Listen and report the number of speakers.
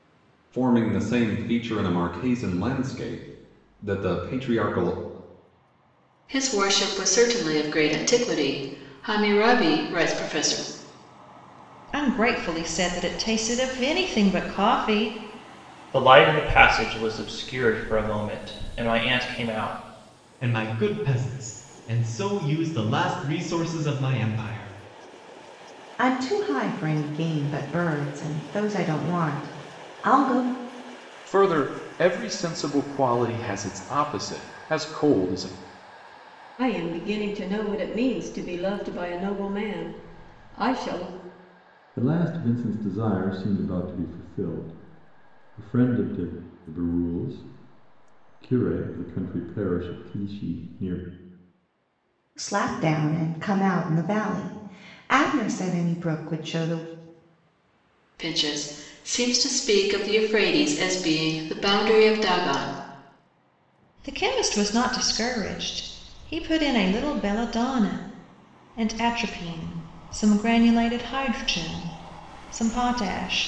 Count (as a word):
nine